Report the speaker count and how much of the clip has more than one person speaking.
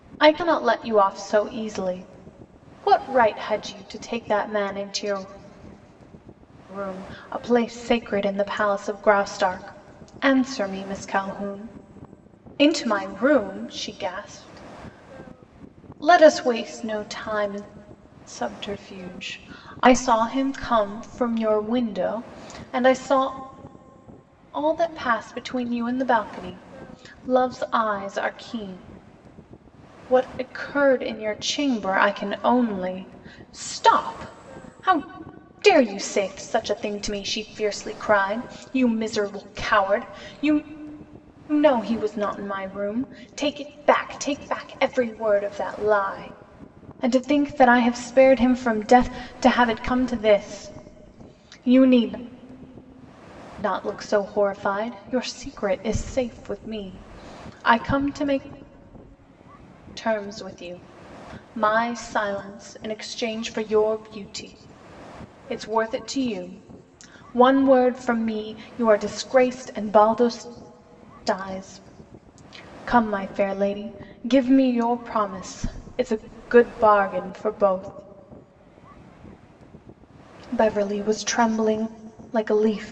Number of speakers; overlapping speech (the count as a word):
one, no overlap